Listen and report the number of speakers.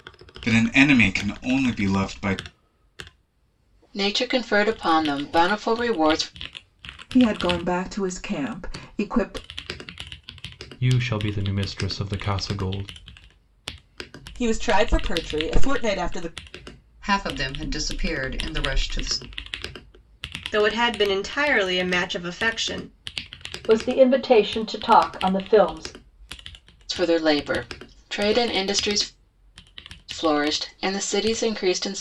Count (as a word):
eight